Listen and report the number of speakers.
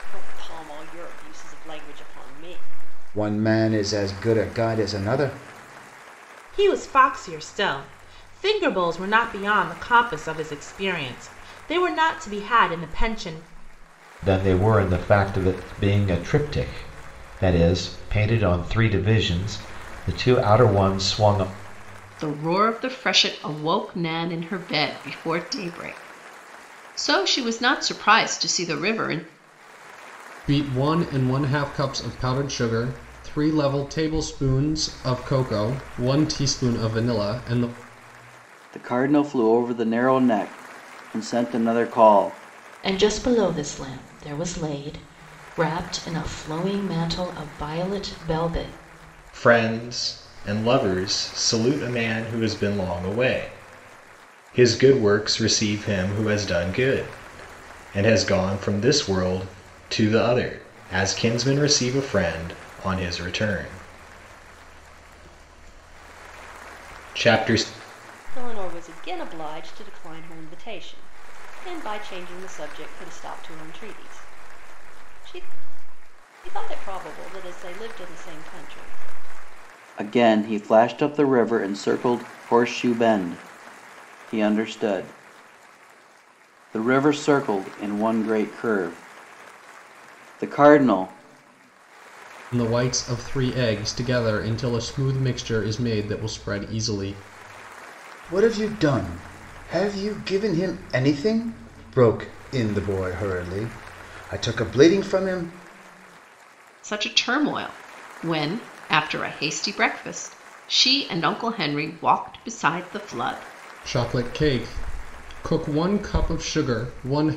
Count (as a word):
nine